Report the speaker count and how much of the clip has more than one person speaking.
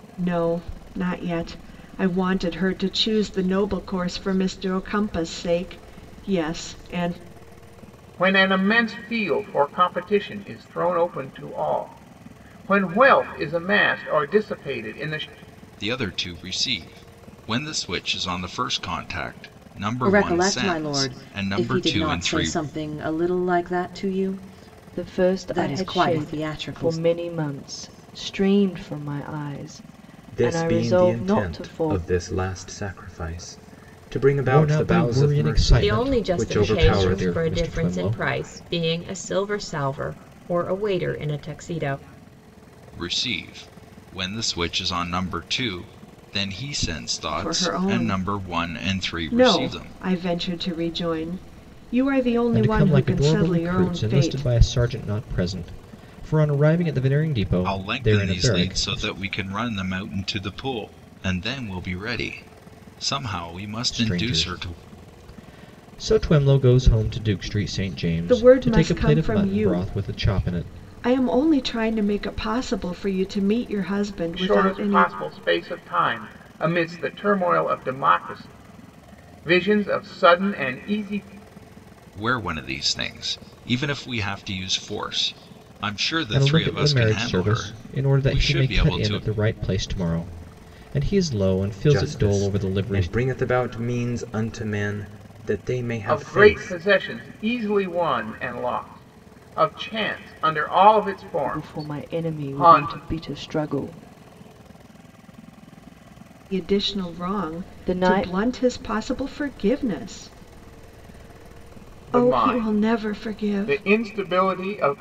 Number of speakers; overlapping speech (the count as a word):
eight, about 27%